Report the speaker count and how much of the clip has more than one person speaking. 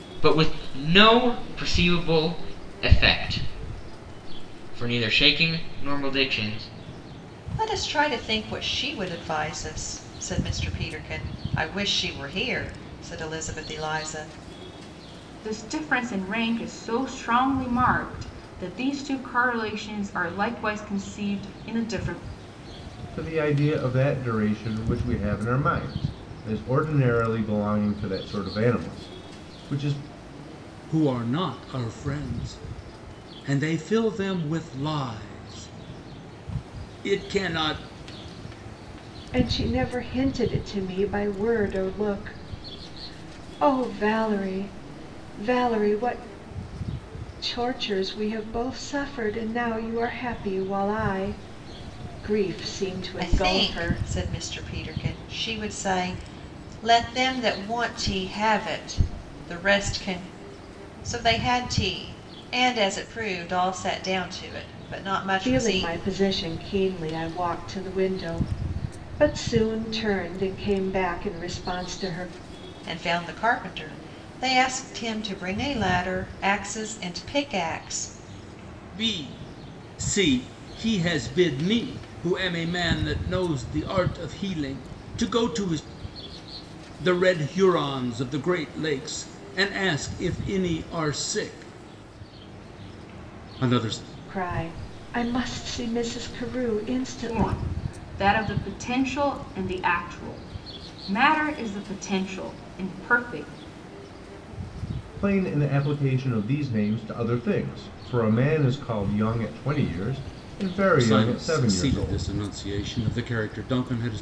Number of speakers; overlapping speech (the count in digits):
6, about 3%